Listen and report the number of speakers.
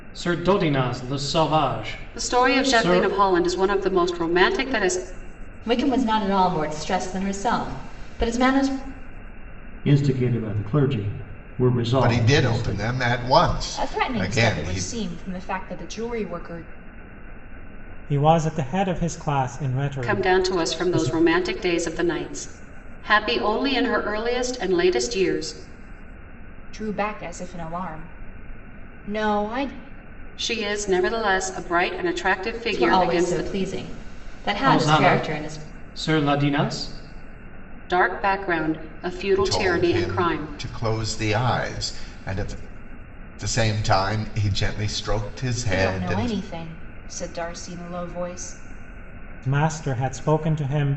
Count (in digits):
7